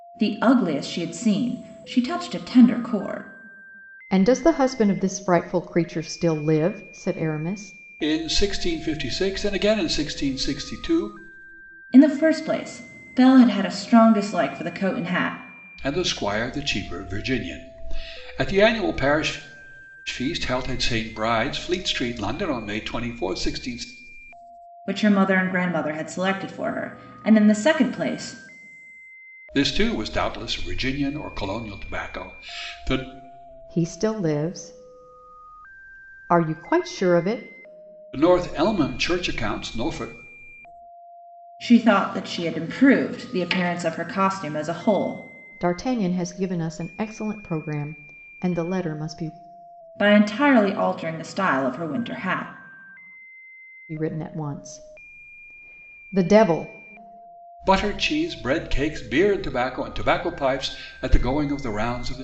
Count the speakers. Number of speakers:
3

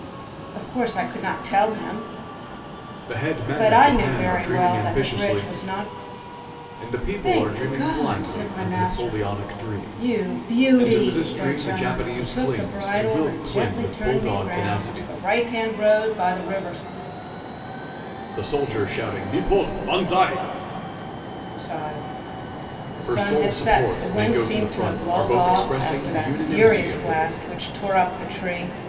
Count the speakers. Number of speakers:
2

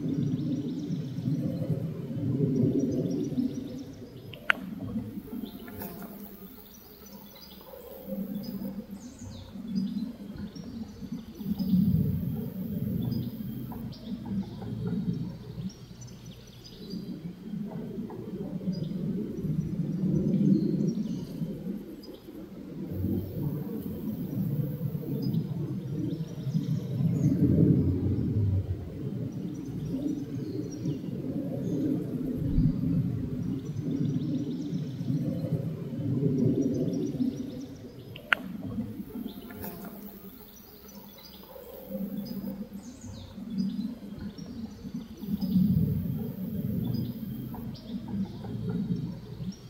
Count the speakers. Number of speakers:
0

